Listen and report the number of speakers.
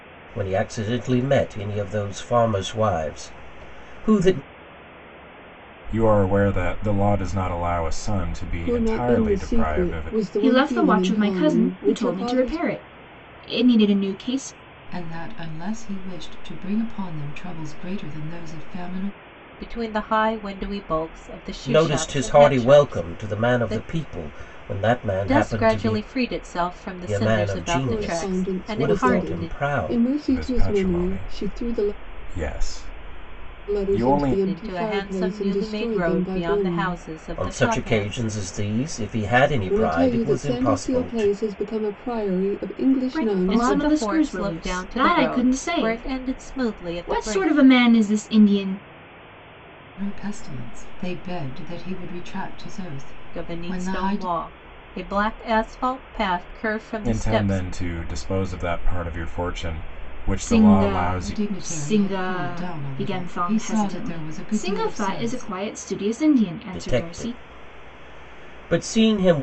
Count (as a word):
six